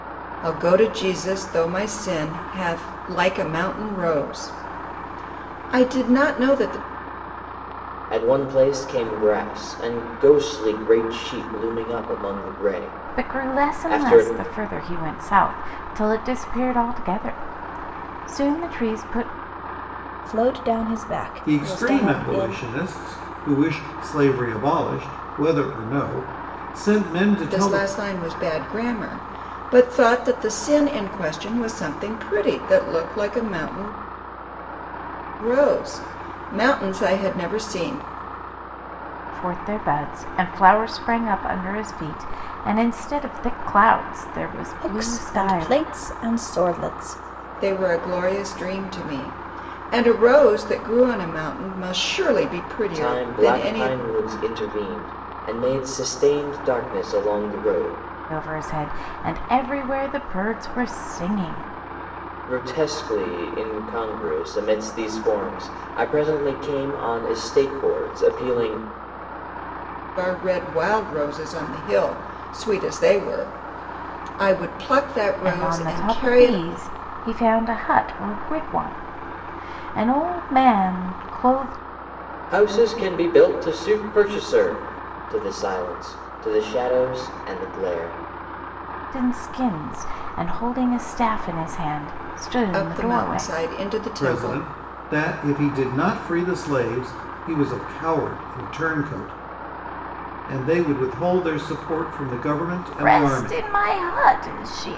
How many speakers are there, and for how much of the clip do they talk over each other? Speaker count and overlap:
5, about 8%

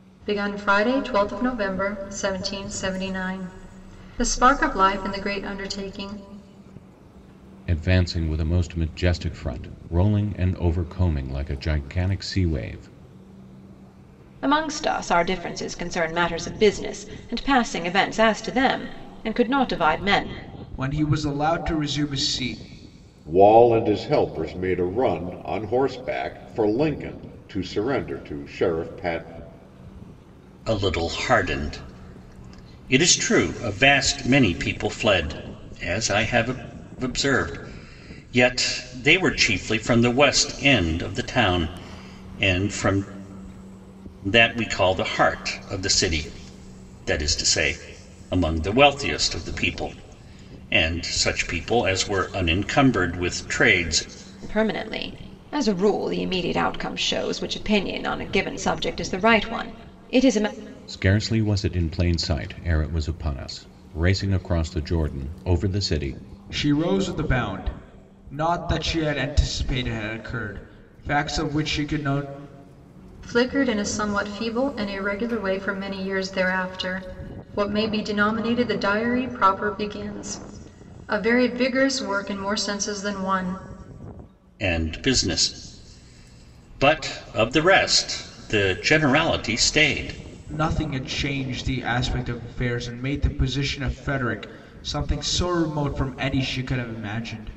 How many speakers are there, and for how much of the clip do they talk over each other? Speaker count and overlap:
6, no overlap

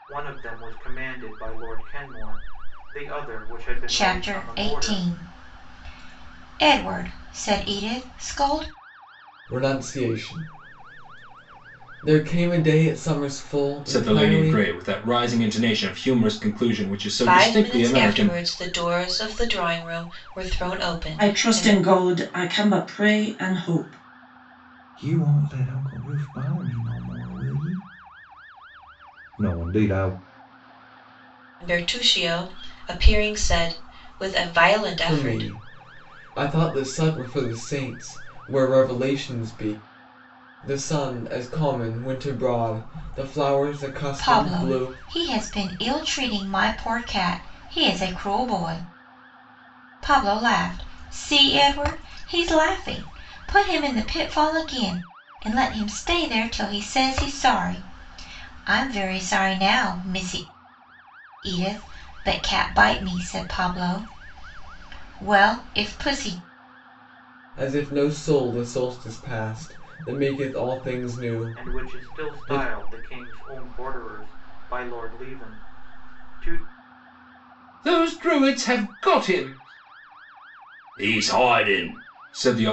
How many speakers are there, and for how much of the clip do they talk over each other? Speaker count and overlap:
7, about 7%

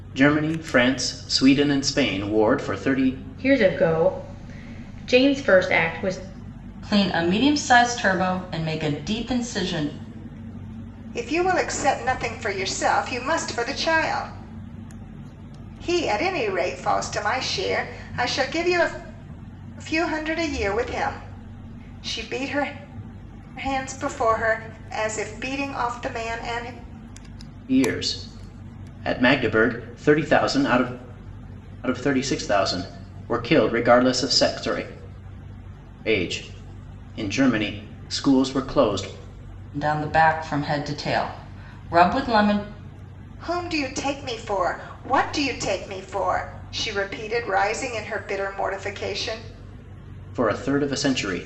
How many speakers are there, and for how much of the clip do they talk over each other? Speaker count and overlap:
4, no overlap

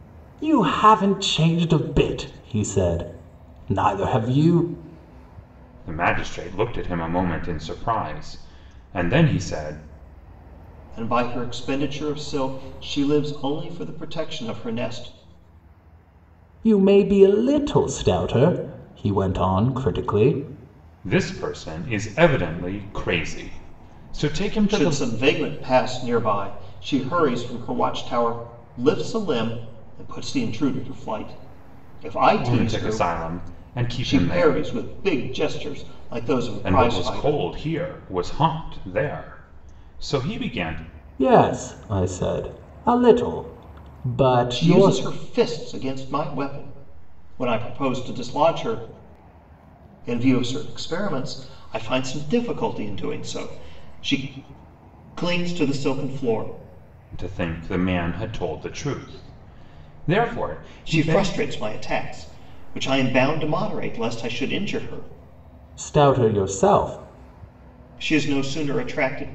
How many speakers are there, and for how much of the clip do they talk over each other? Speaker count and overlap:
3, about 5%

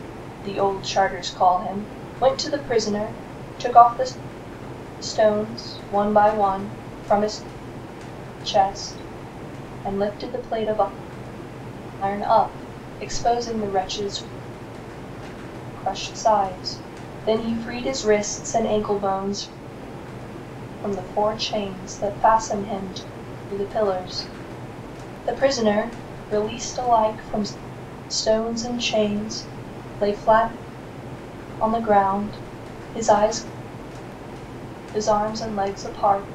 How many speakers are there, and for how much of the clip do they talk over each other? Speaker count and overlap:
1, no overlap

